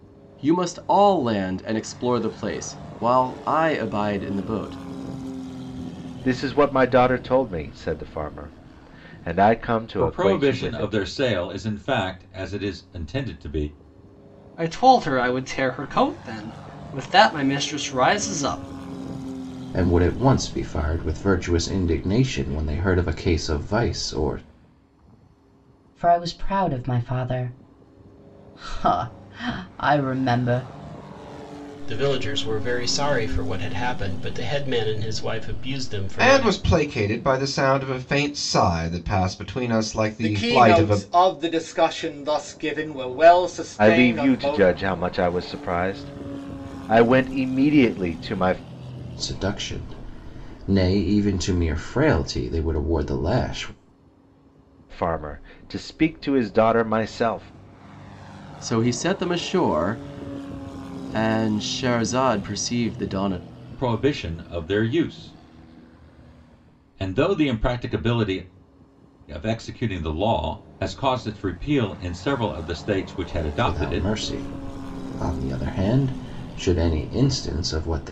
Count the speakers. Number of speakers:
nine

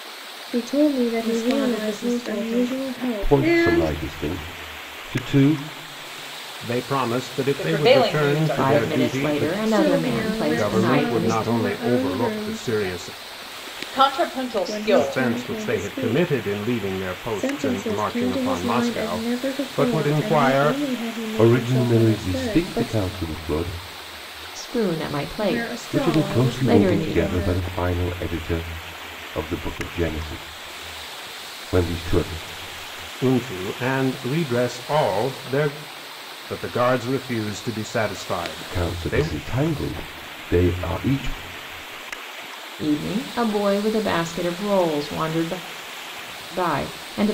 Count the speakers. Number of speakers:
six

